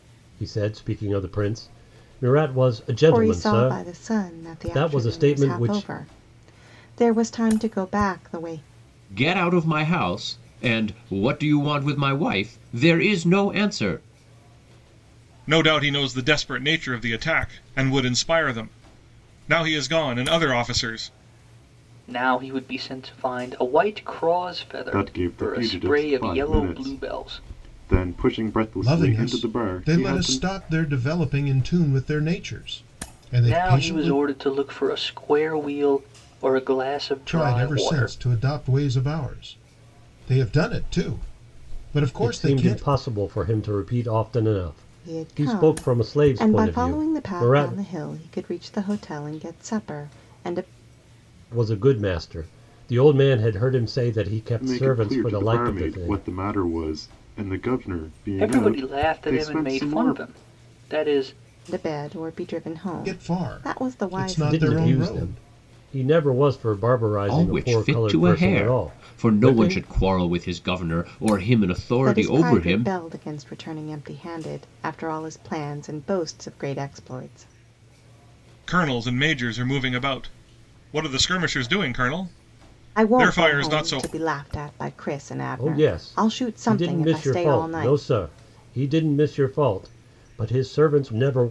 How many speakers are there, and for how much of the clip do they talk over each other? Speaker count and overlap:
7, about 28%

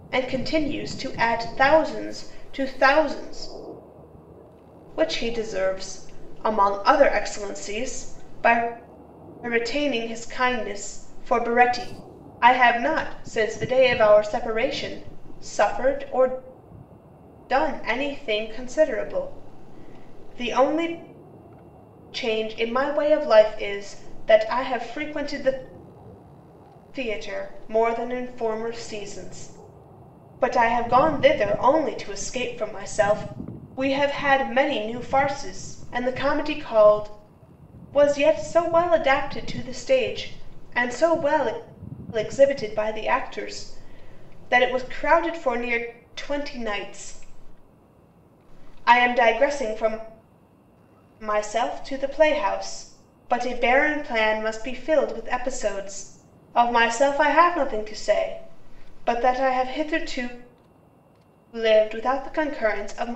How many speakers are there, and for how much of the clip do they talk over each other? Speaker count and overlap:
1, no overlap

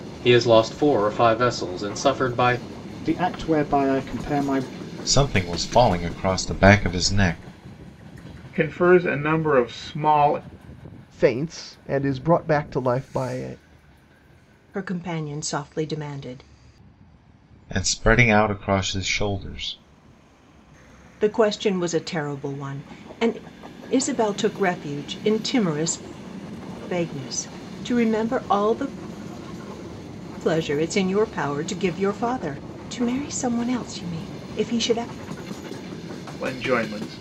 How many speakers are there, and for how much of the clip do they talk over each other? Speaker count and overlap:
6, no overlap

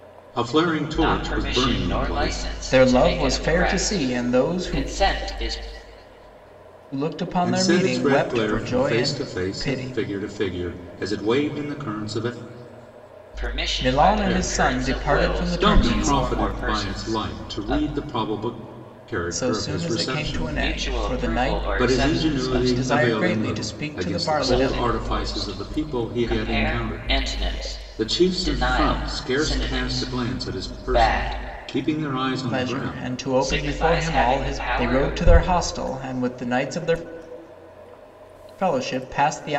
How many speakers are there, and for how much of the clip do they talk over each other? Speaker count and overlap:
3, about 61%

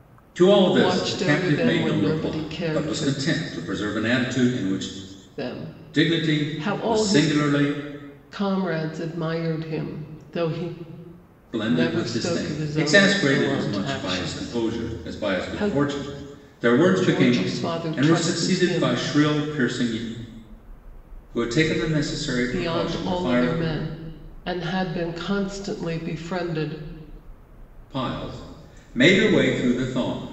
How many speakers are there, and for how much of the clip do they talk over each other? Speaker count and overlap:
2, about 35%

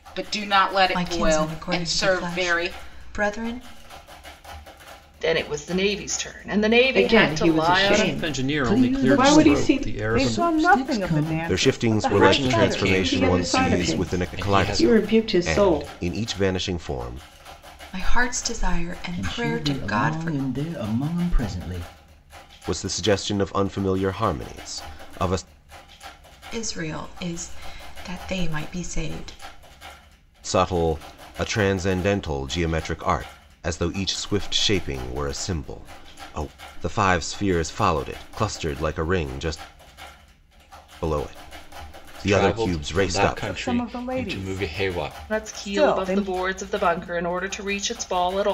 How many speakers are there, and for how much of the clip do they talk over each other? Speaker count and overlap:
9, about 33%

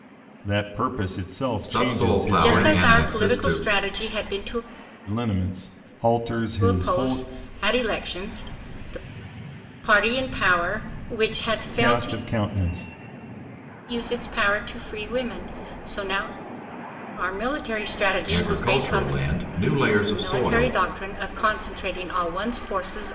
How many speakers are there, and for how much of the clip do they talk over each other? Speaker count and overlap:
3, about 20%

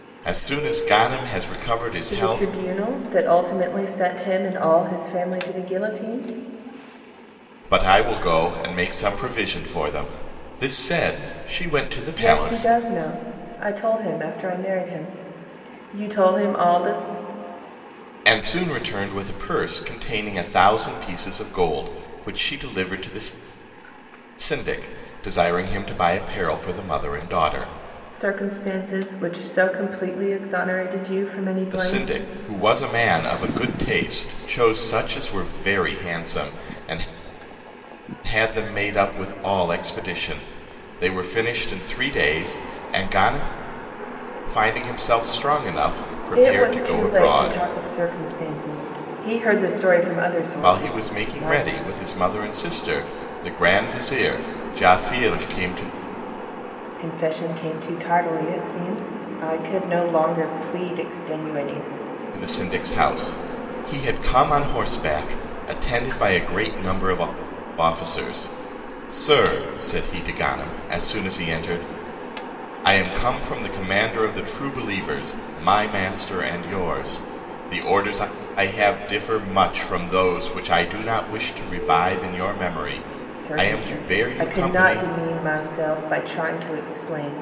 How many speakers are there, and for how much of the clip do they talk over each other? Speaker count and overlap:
2, about 6%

